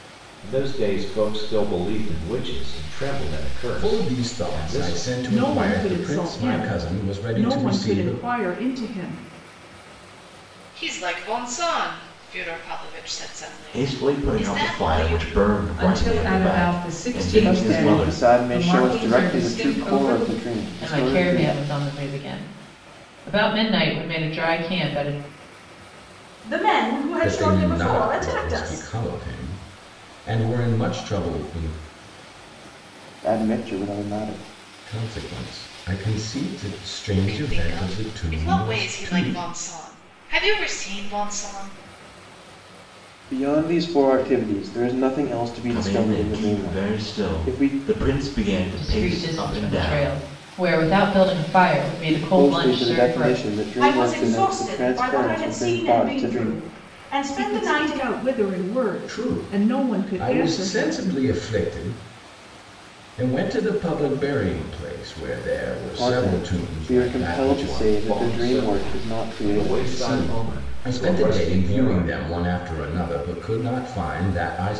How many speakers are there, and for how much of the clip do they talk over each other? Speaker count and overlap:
nine, about 43%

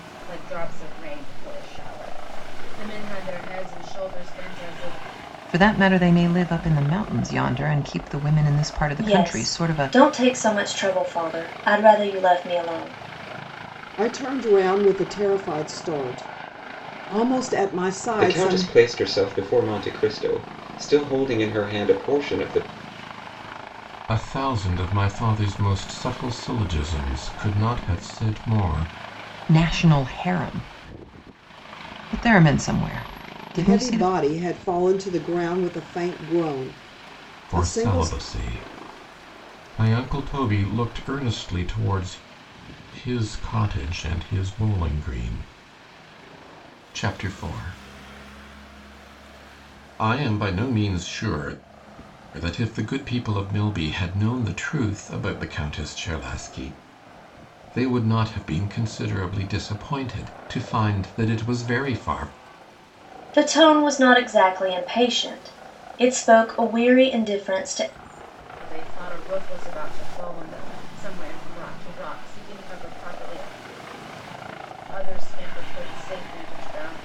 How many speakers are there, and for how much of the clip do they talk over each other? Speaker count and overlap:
six, about 4%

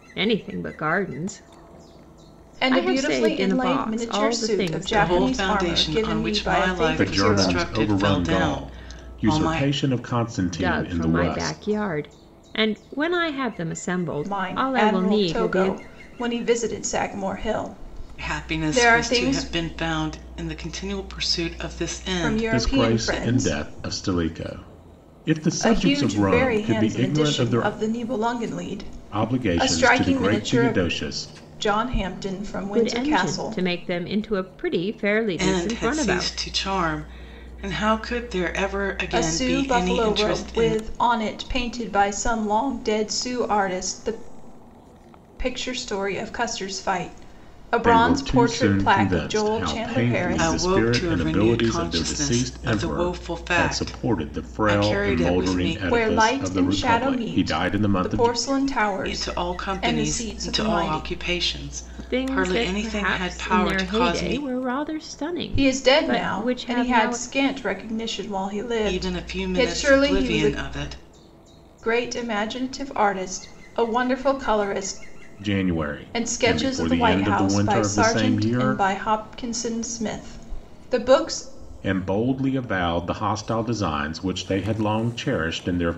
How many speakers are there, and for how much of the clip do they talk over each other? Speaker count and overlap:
four, about 47%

